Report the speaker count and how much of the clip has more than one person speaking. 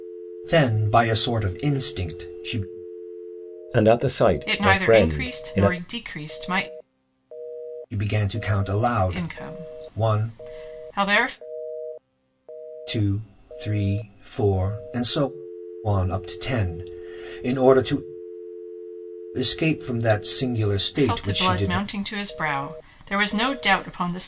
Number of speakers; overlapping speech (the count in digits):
3, about 14%